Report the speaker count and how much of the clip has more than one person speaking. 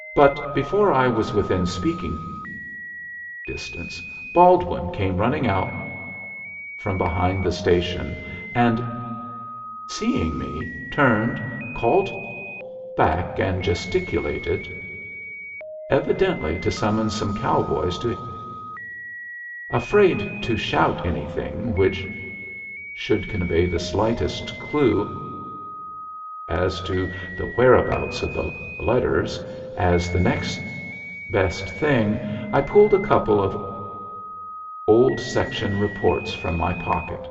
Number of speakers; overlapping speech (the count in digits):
1, no overlap